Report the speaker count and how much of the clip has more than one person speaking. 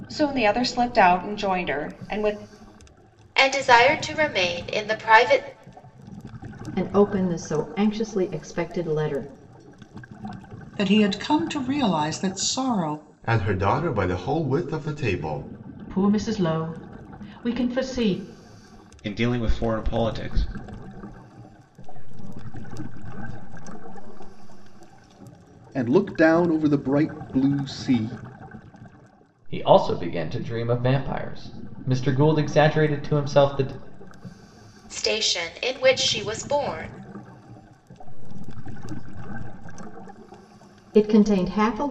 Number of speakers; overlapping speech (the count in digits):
10, no overlap